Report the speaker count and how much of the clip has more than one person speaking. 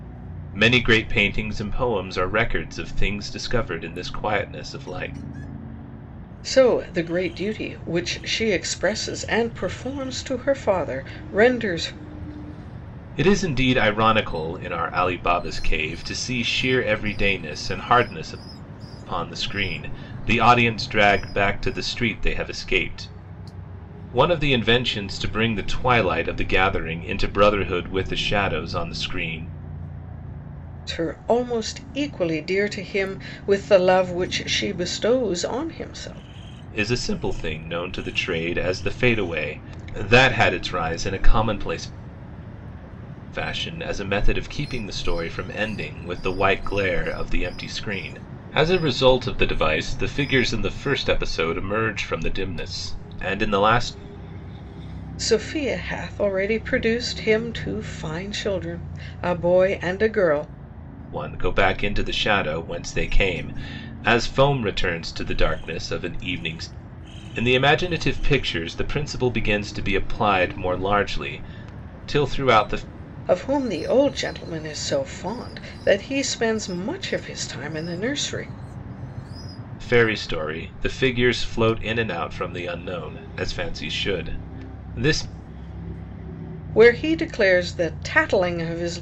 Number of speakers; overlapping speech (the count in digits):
2, no overlap